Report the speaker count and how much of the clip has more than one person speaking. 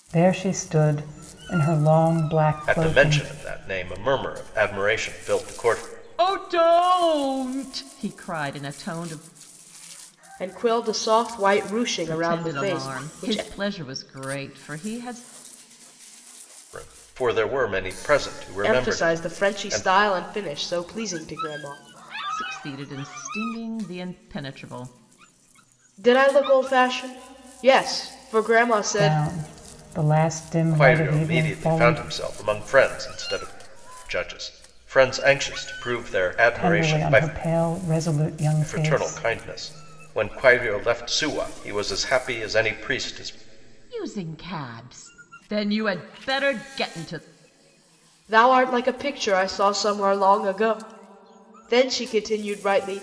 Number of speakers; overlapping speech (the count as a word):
four, about 12%